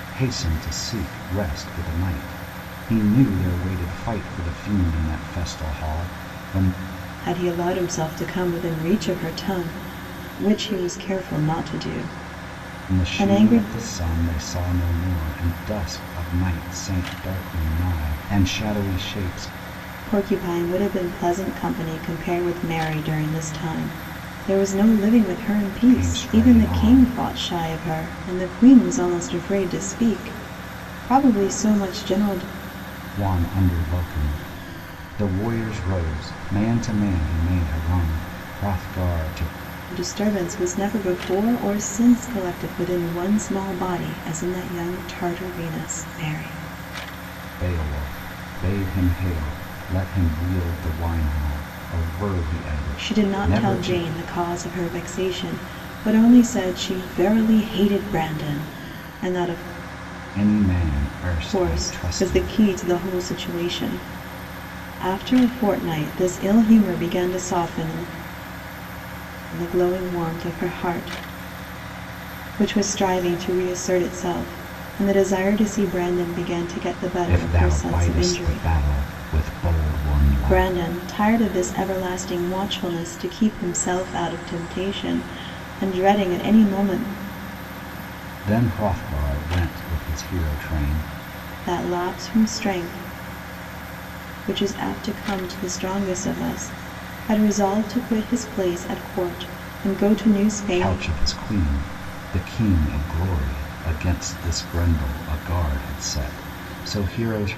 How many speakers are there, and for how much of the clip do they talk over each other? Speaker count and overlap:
2, about 6%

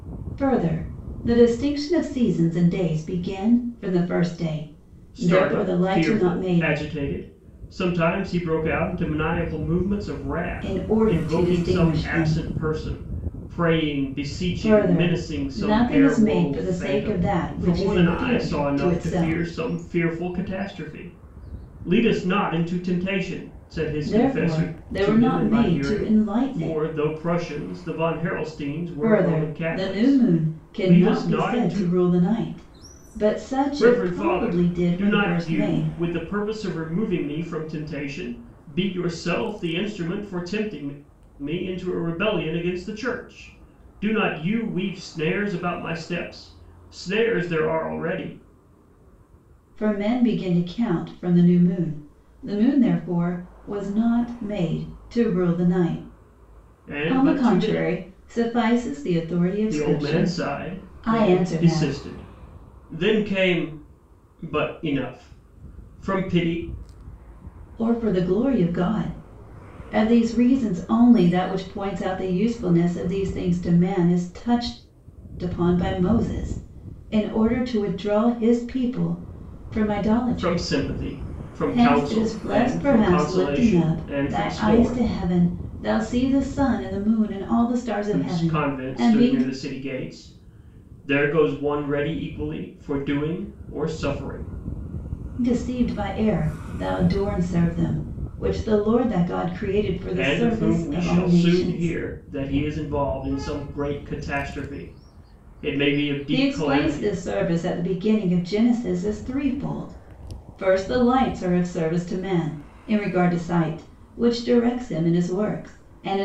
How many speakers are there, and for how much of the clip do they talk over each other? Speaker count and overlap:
2, about 24%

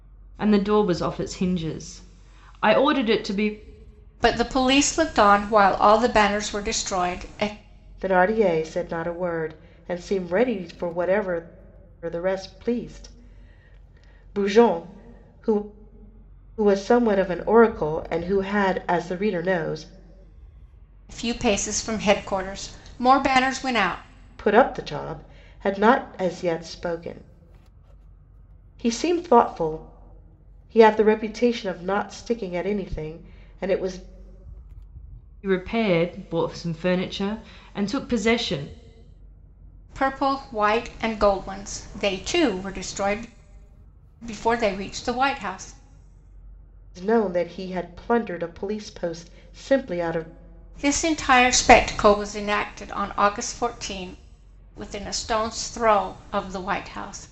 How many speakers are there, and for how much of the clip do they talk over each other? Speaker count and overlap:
3, no overlap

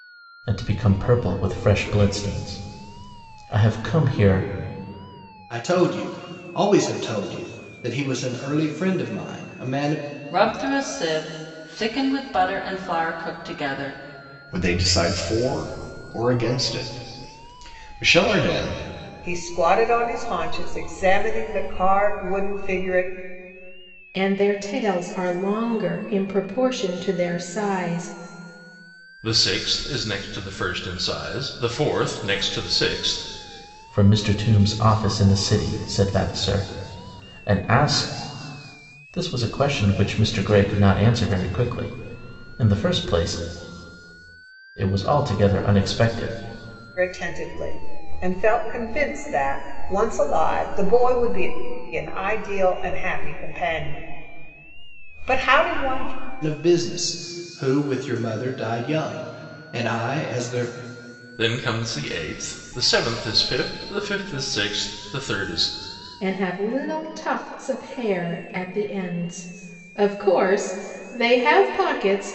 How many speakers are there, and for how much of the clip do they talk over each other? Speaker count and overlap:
7, no overlap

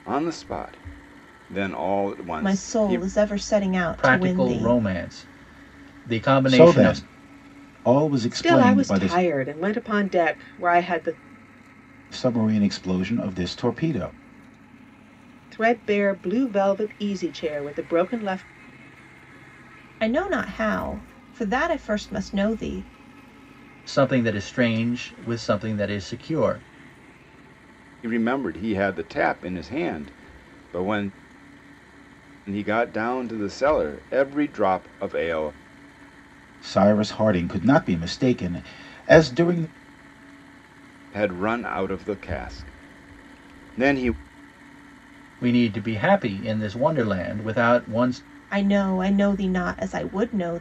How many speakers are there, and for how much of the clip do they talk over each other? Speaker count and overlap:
5, about 6%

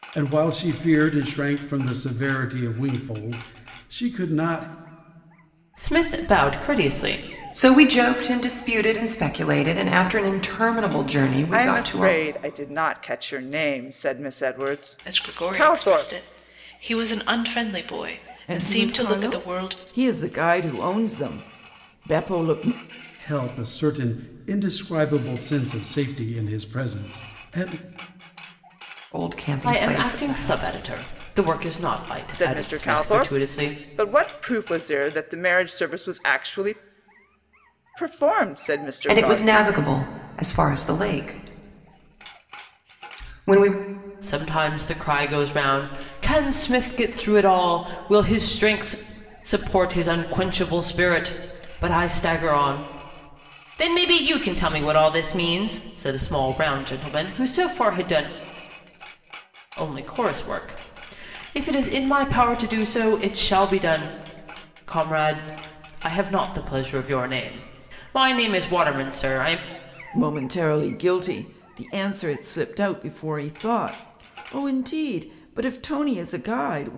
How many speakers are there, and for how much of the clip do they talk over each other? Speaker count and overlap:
6, about 8%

